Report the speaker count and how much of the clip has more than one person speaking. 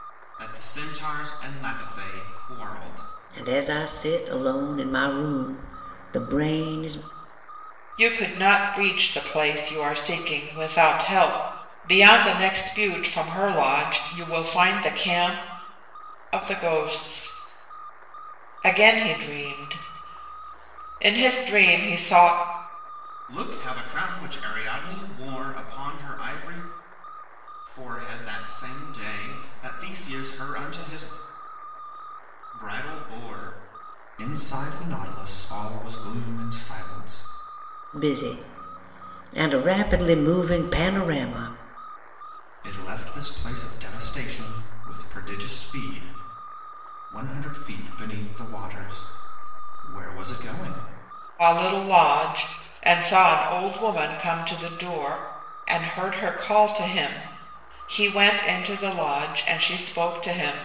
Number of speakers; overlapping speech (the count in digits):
3, no overlap